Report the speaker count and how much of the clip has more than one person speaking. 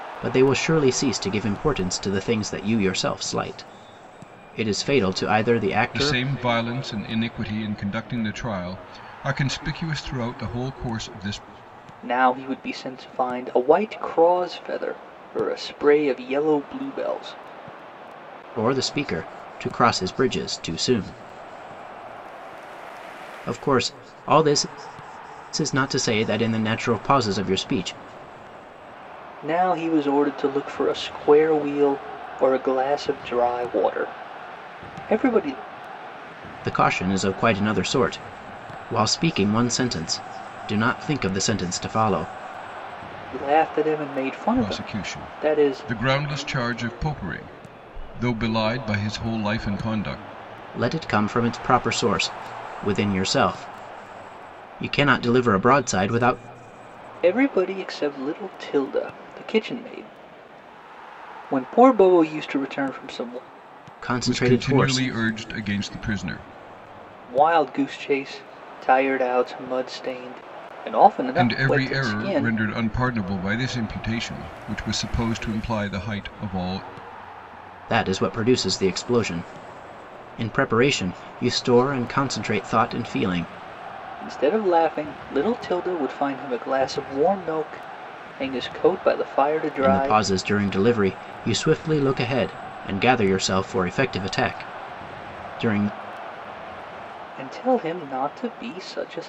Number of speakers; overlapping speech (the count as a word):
three, about 4%